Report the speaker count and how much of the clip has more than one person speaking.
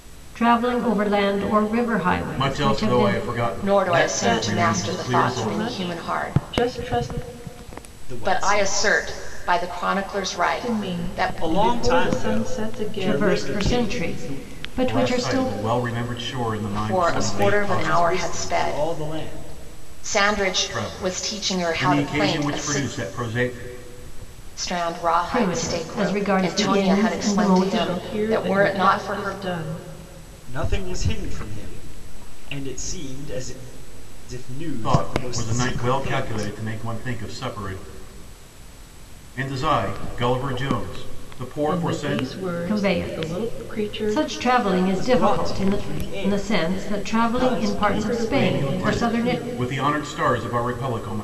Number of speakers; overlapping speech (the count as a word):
five, about 51%